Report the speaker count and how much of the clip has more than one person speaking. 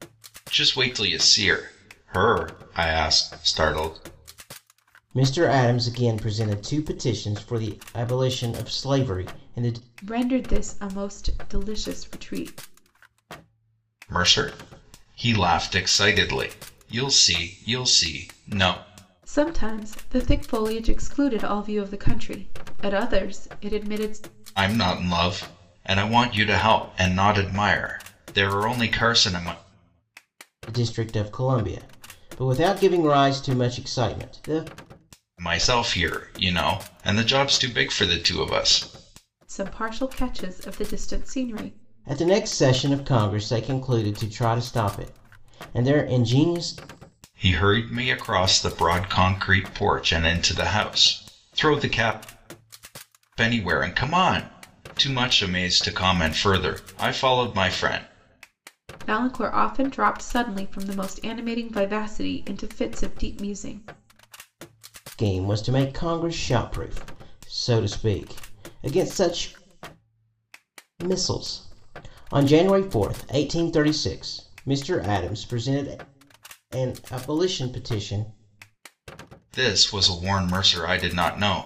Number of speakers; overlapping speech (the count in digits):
3, no overlap